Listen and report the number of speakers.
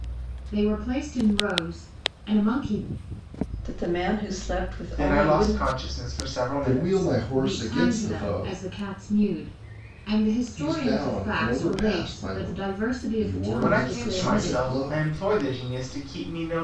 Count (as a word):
four